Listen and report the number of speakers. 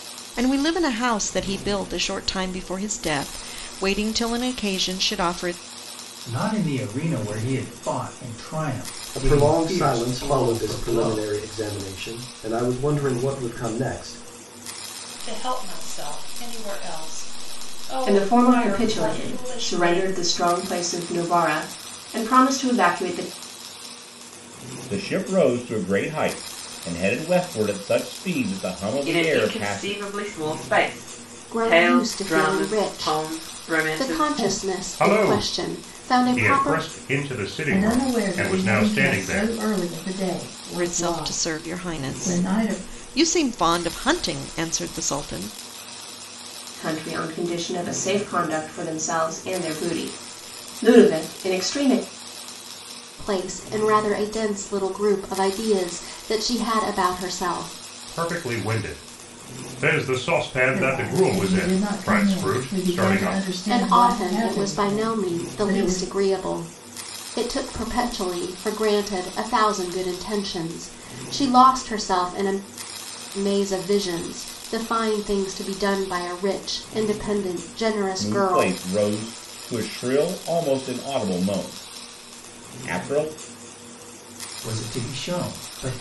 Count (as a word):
ten